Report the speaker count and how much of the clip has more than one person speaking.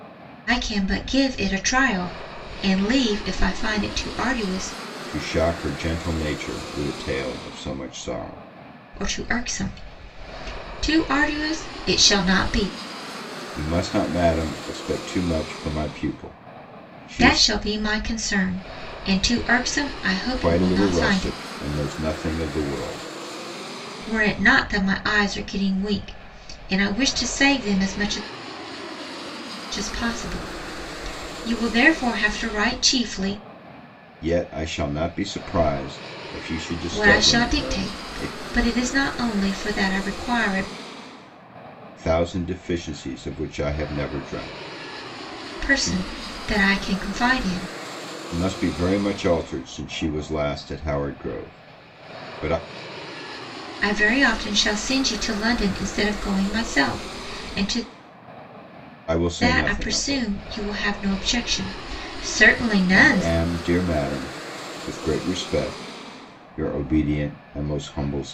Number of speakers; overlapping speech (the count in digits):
2, about 7%